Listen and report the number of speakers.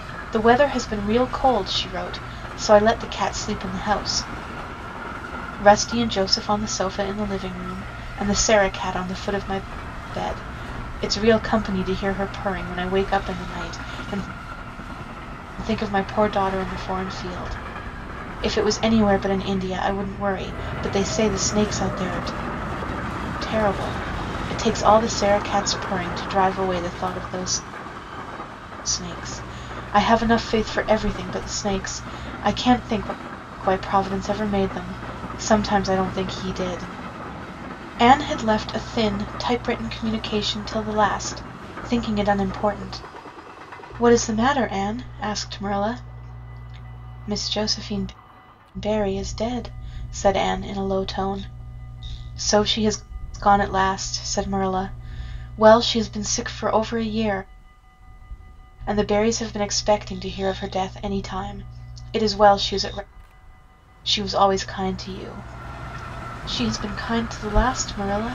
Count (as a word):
one